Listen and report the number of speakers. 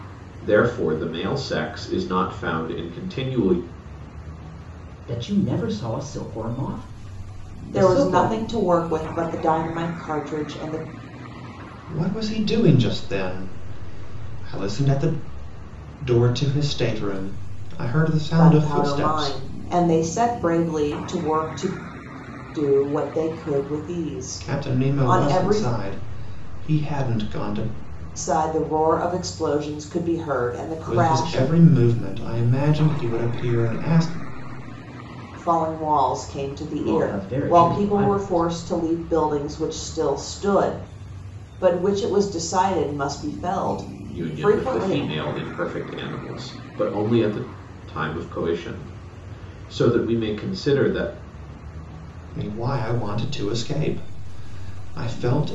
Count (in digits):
4